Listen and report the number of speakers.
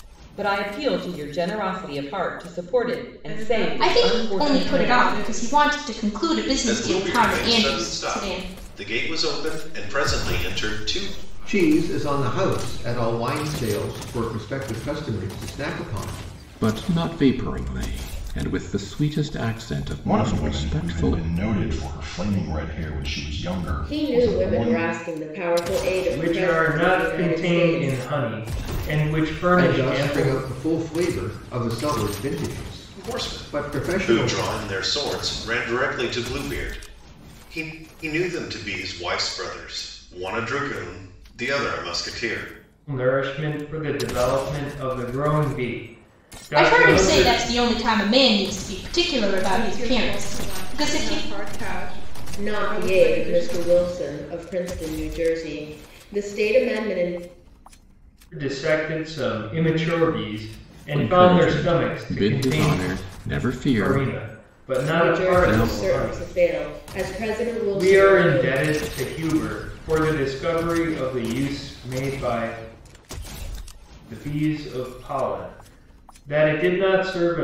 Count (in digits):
10